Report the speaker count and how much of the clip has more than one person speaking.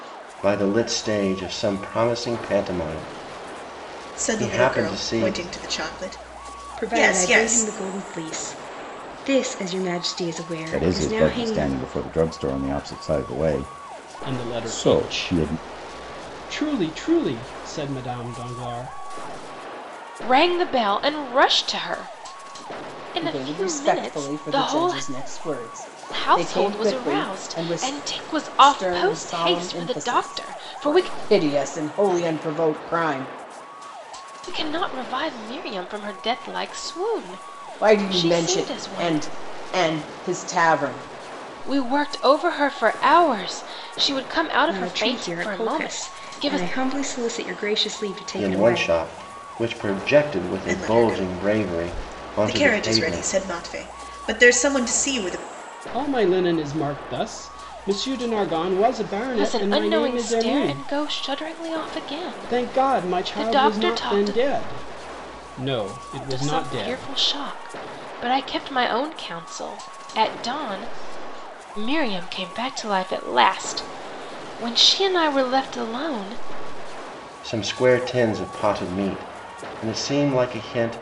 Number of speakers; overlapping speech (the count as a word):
seven, about 27%